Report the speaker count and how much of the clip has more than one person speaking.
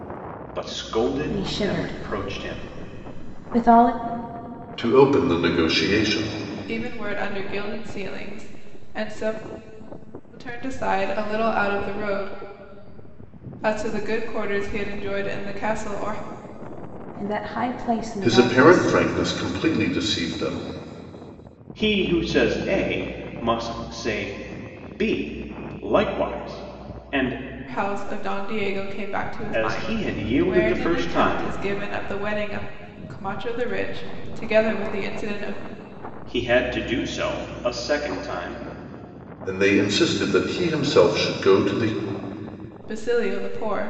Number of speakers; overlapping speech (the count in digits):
4, about 9%